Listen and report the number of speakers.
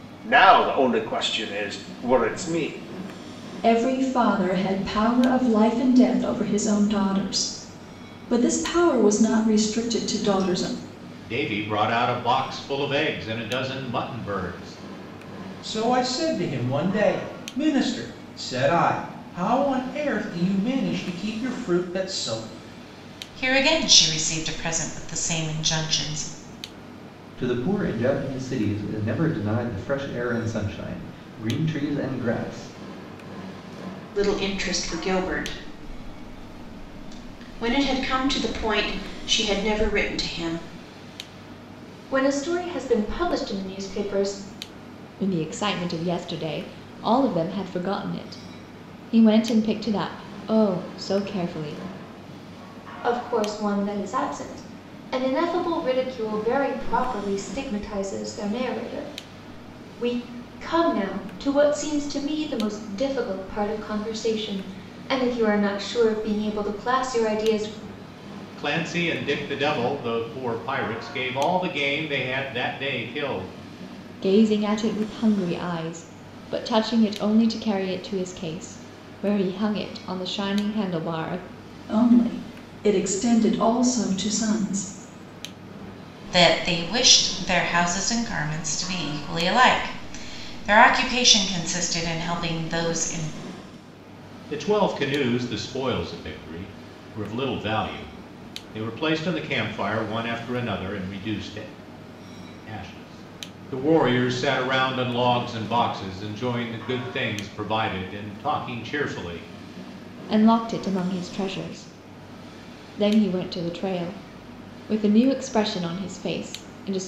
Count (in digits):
9